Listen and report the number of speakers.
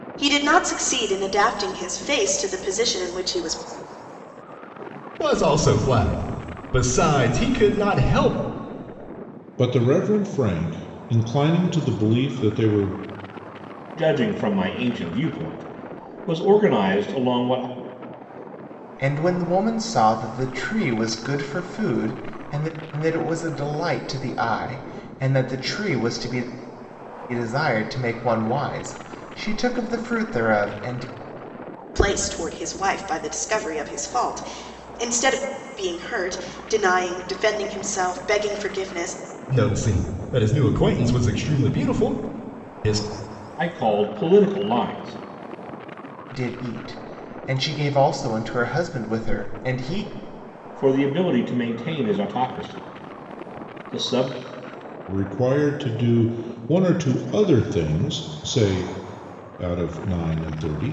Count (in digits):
5